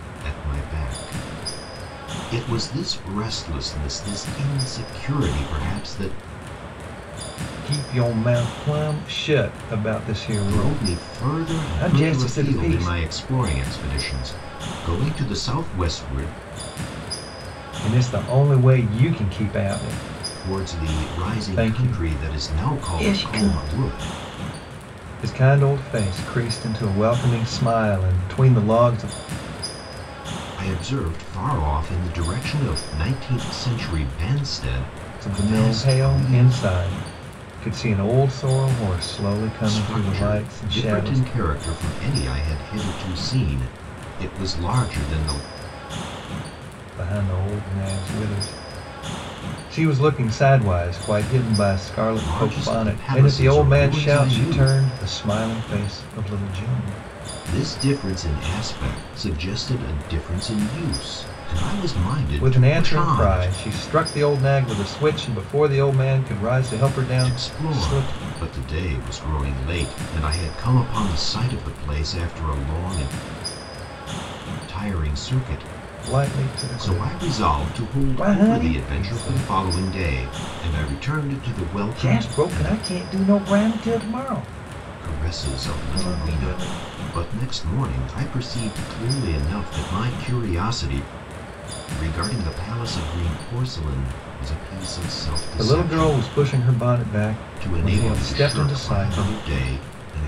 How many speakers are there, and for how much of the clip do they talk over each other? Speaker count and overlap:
two, about 21%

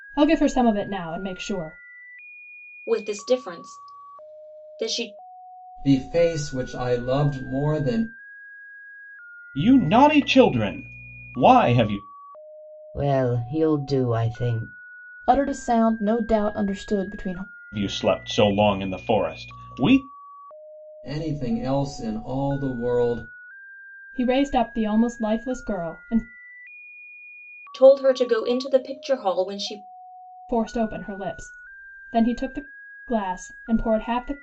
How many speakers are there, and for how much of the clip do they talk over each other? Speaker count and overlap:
six, no overlap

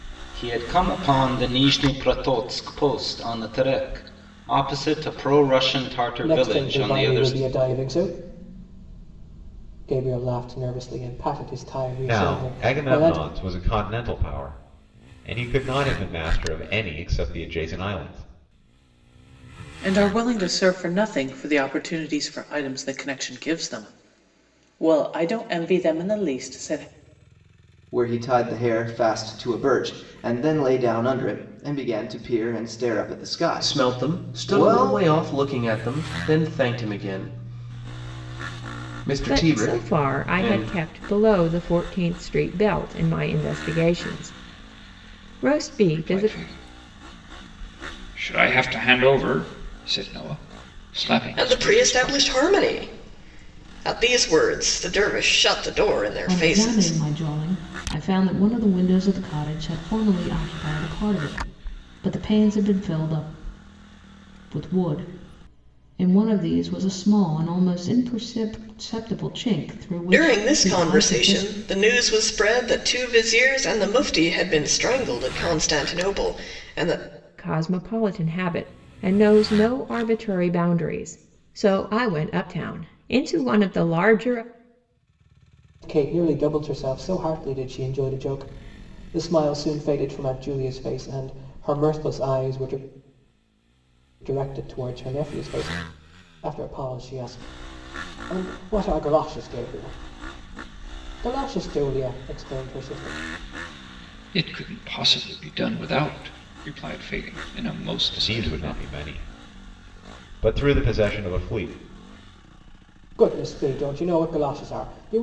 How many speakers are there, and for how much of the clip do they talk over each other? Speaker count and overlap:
ten, about 9%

